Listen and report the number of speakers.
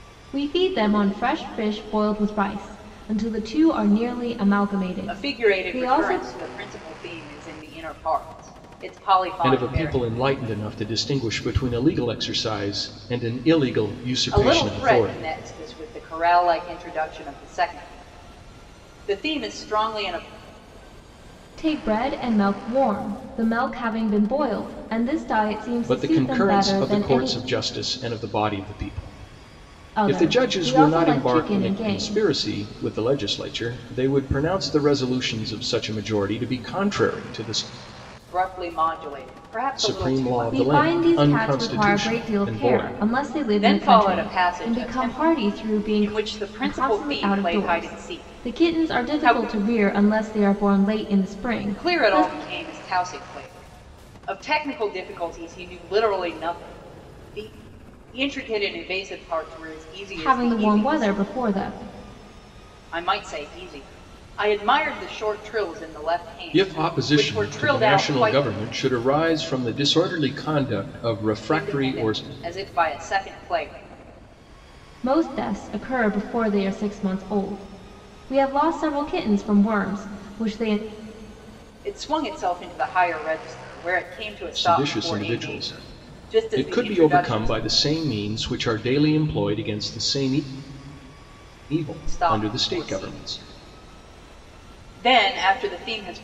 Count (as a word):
three